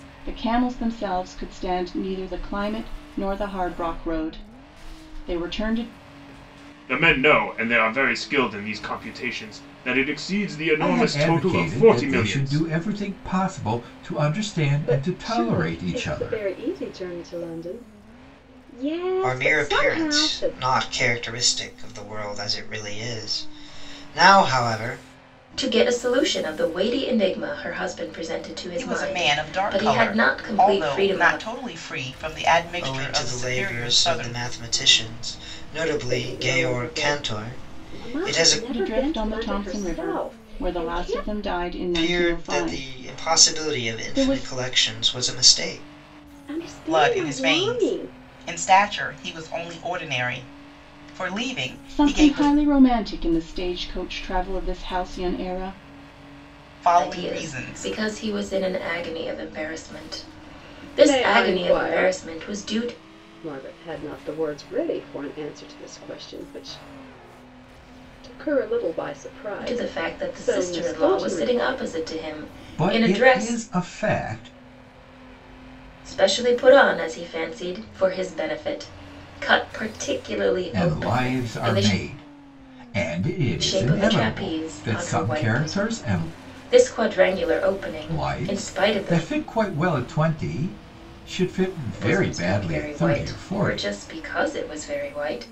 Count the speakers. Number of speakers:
seven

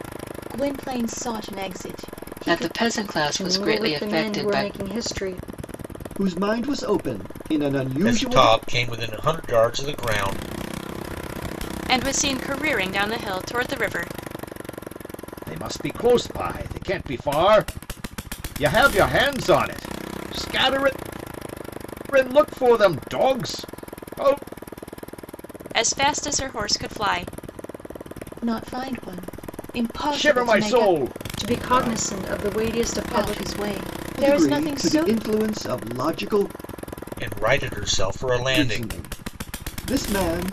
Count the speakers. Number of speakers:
seven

